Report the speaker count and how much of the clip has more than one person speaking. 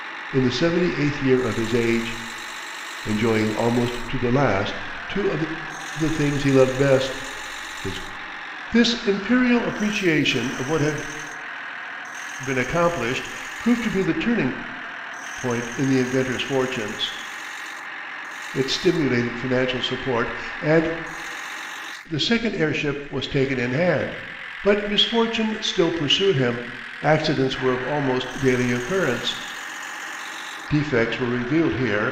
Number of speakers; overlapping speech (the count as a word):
one, no overlap